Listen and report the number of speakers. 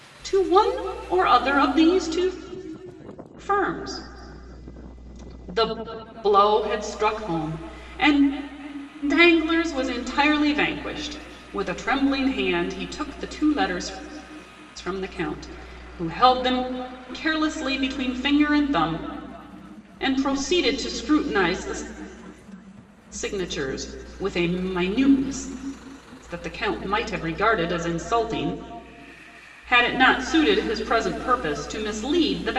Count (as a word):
one